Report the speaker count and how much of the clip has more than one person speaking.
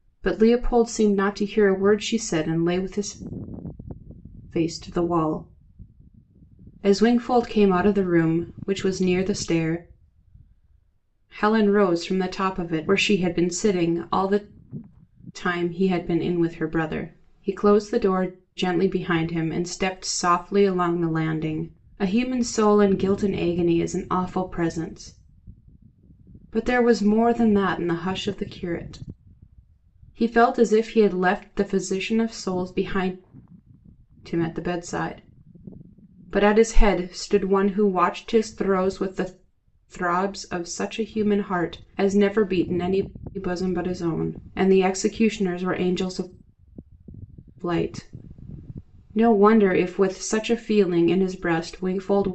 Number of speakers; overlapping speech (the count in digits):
1, no overlap